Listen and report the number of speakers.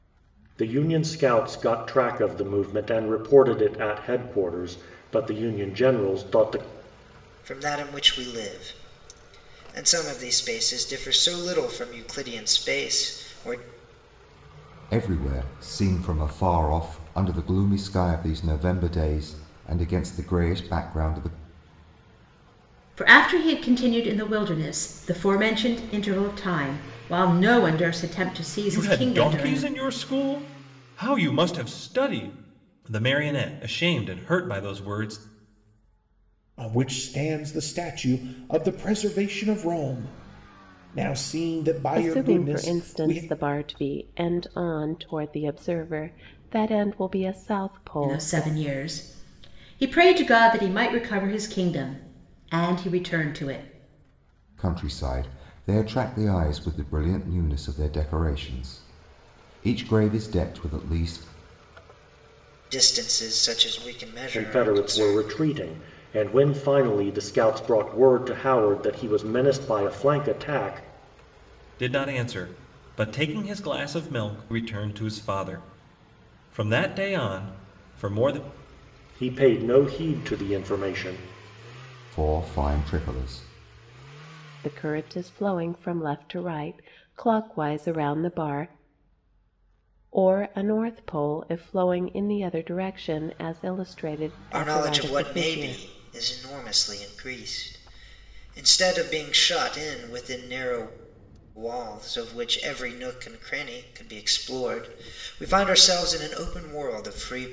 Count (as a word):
seven